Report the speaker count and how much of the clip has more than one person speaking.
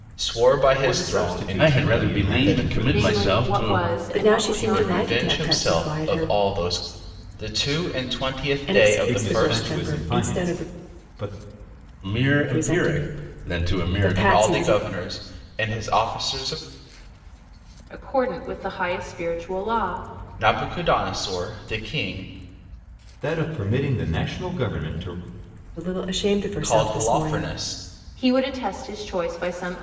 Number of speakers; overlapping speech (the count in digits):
5, about 36%